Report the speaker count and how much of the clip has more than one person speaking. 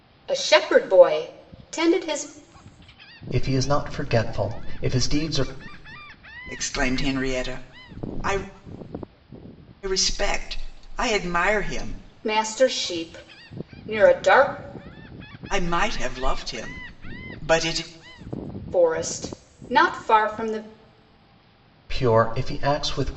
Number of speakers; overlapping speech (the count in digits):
3, no overlap